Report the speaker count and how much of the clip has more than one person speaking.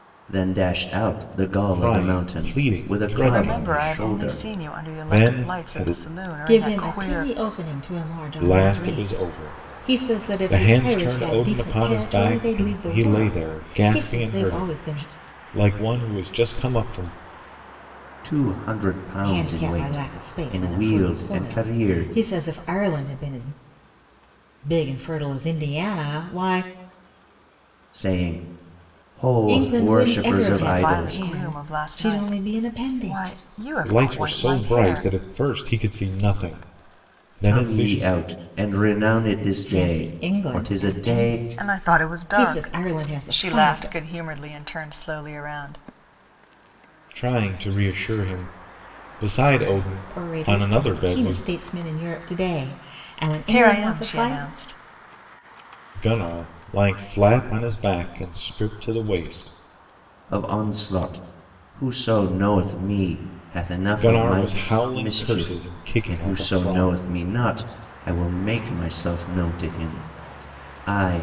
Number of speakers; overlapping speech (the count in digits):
4, about 42%